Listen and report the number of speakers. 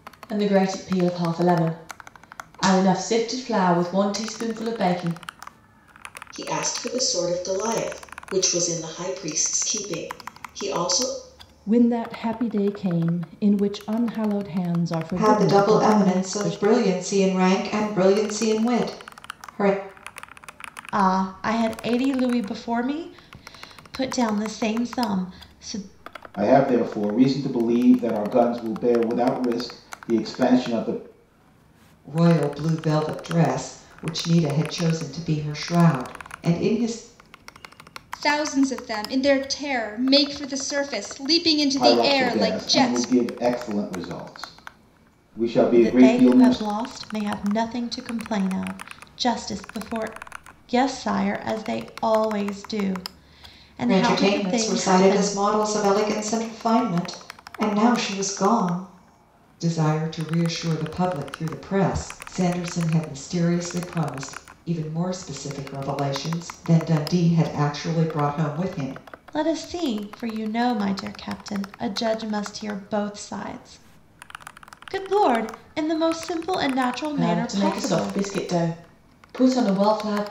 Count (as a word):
eight